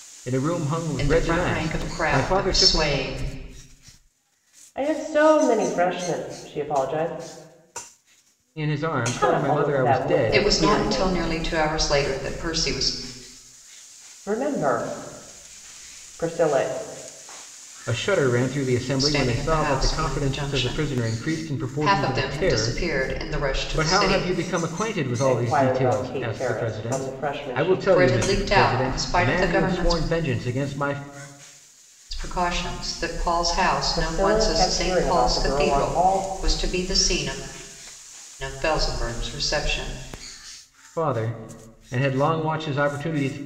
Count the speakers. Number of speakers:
3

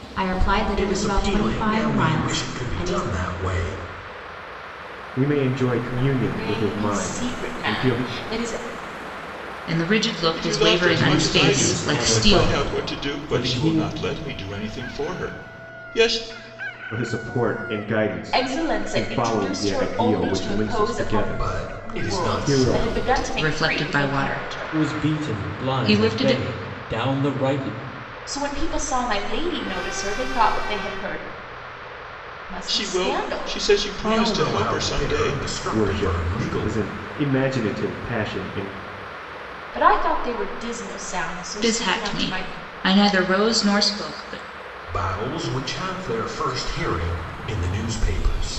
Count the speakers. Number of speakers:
7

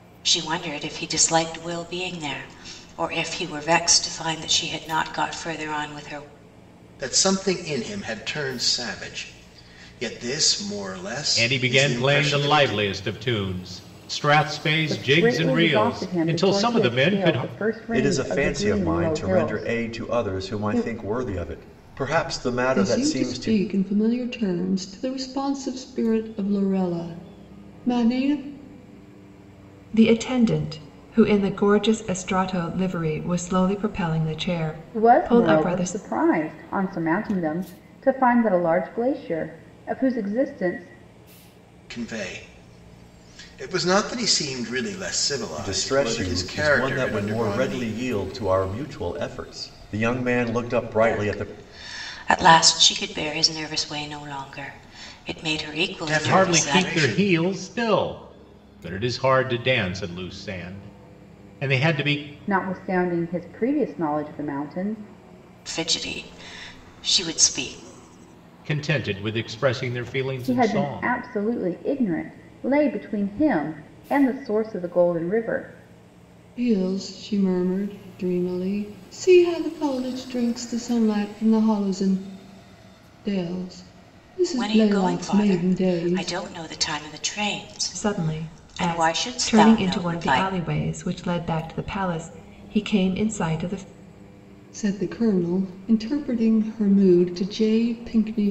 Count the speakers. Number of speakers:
7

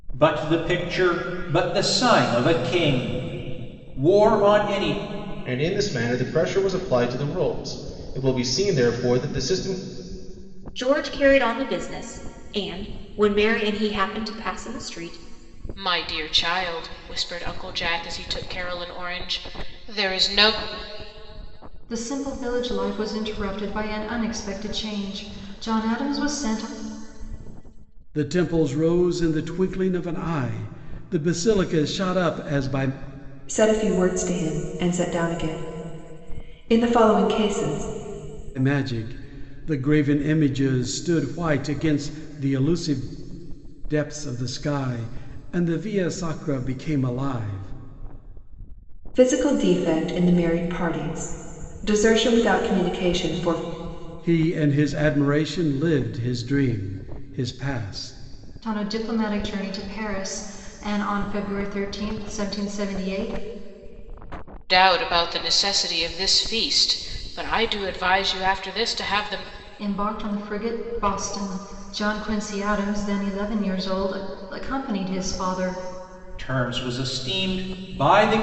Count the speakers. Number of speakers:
7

